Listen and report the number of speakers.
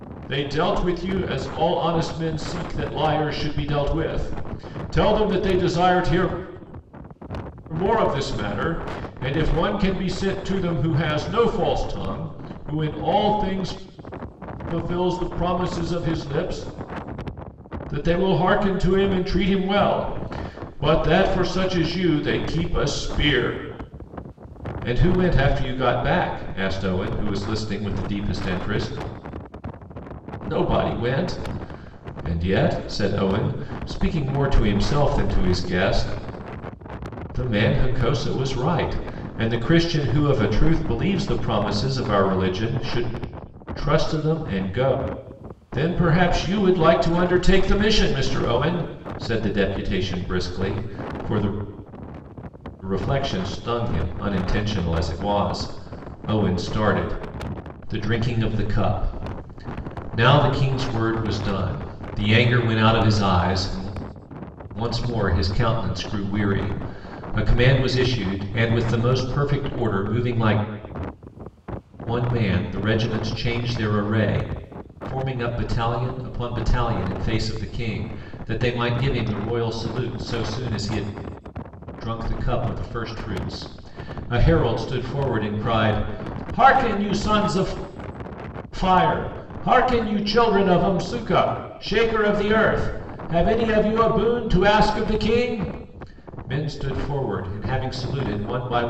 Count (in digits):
1